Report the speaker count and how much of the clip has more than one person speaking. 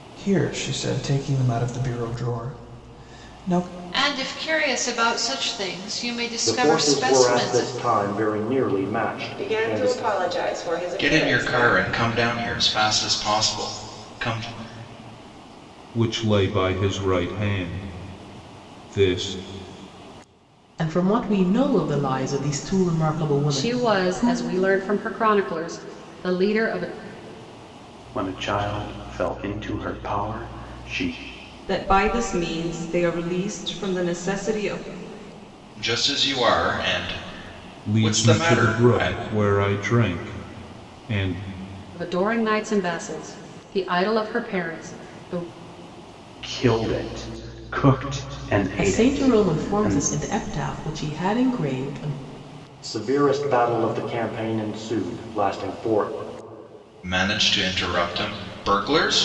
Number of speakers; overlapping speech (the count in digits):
10, about 11%